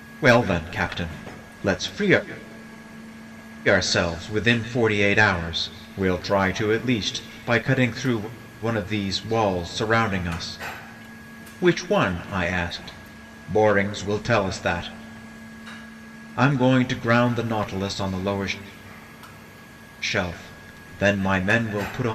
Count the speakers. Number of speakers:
one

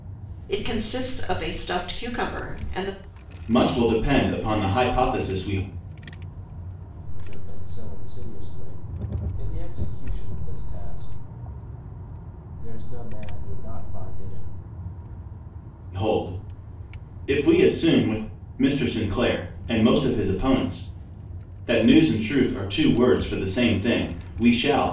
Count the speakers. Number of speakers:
three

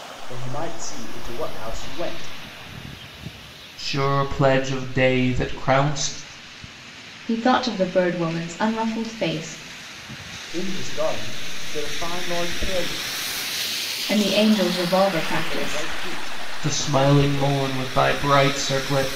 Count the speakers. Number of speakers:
three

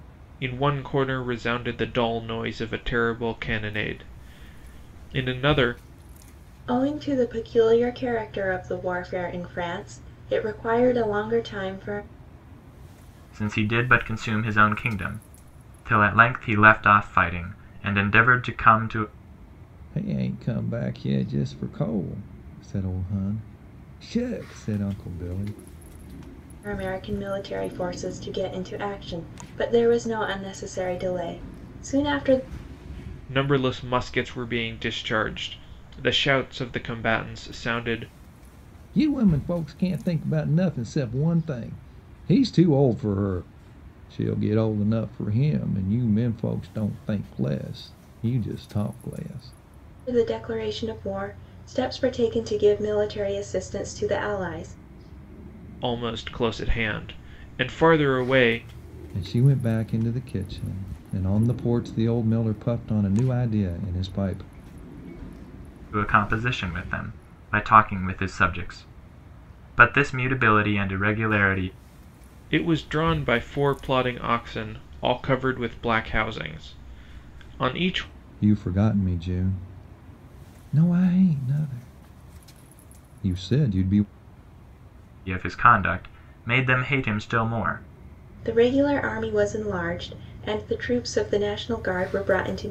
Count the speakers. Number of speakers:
four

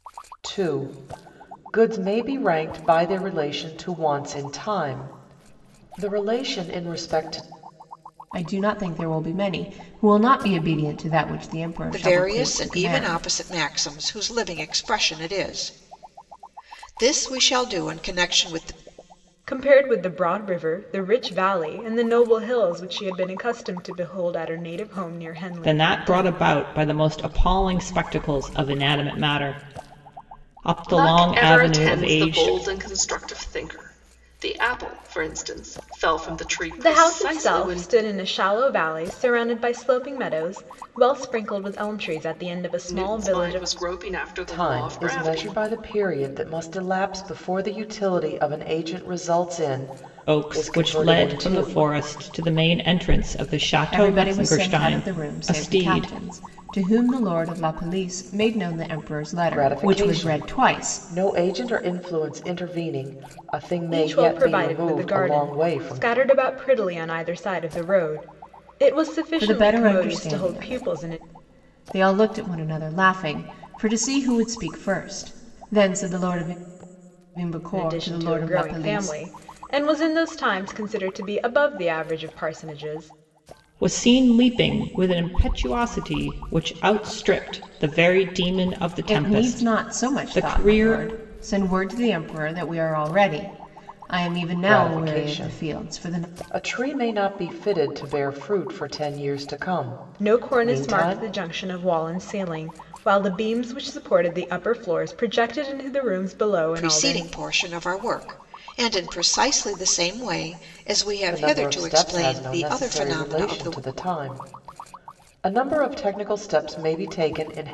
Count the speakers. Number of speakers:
six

